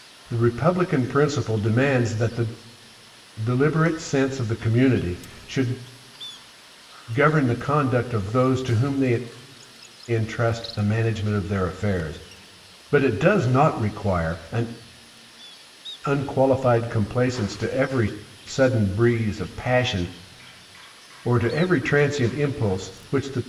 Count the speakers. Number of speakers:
1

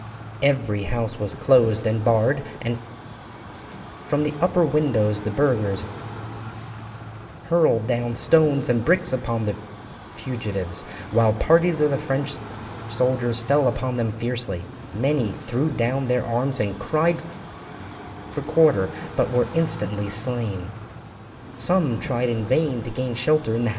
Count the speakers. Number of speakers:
1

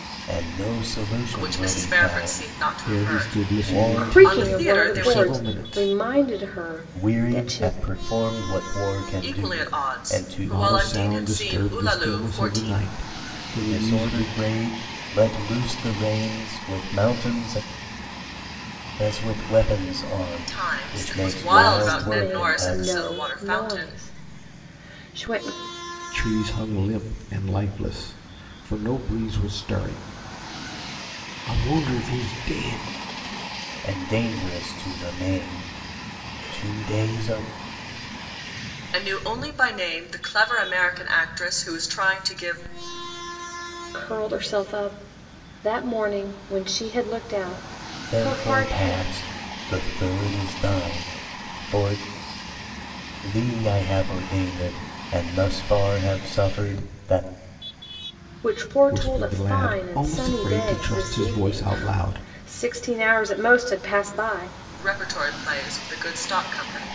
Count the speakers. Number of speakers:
4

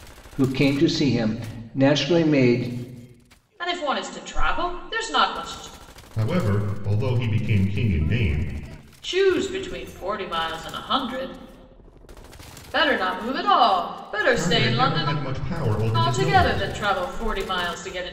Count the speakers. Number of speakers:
3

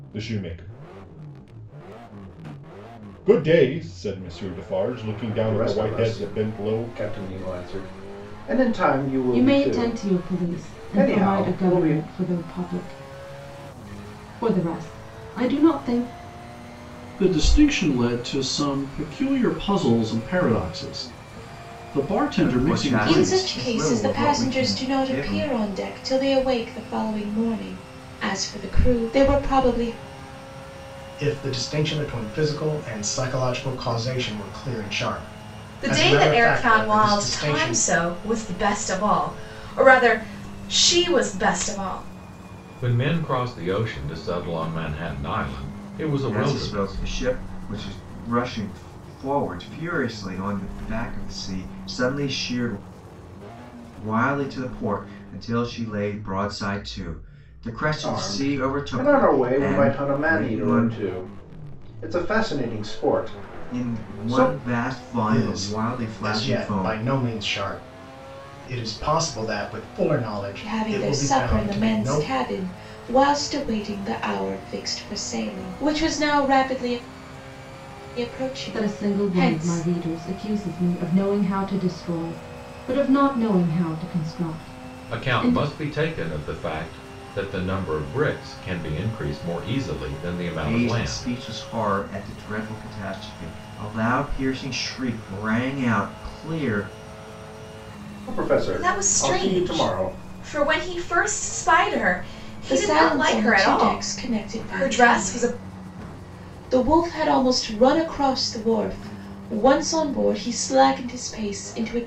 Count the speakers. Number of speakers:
9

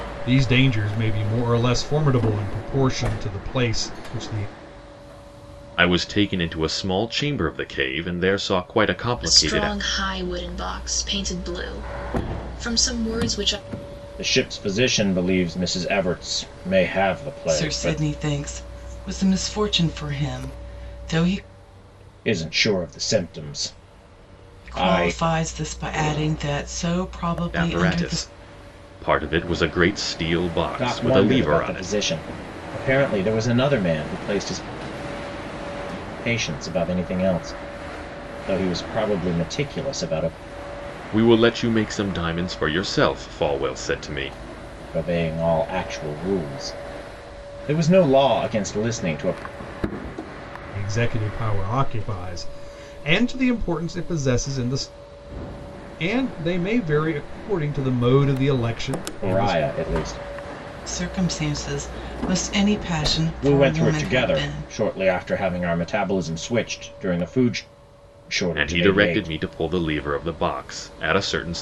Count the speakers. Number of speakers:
5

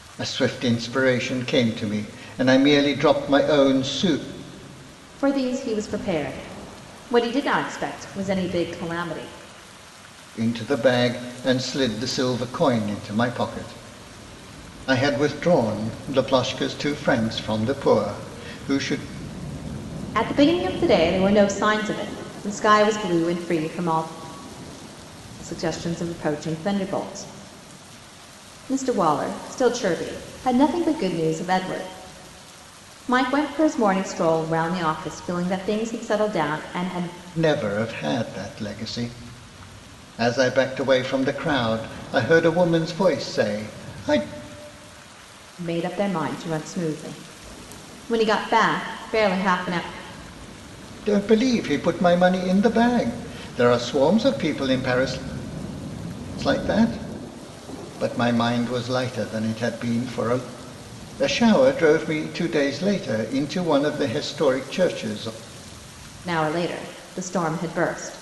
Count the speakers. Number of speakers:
2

